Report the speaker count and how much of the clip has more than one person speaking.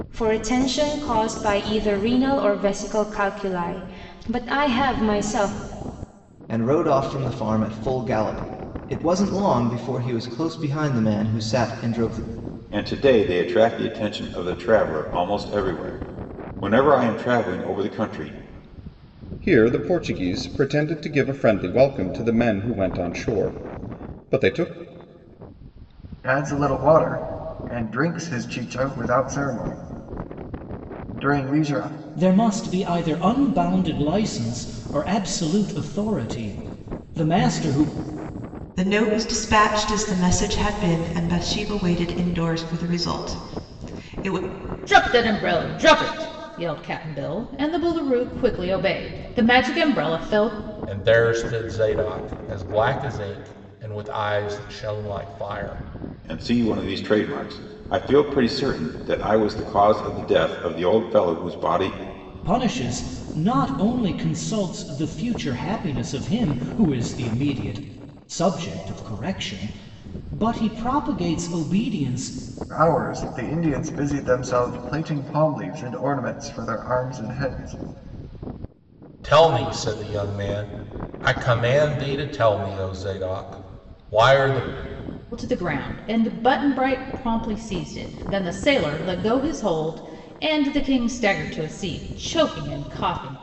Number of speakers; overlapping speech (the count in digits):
9, no overlap